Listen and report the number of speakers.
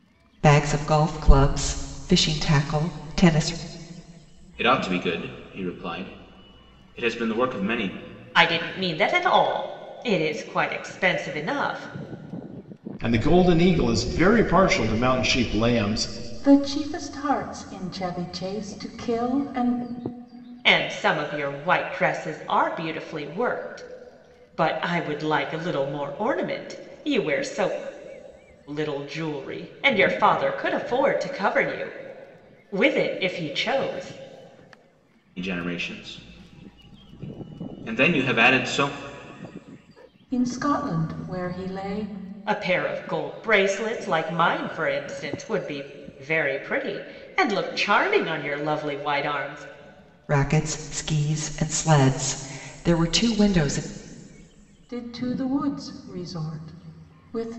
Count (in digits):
5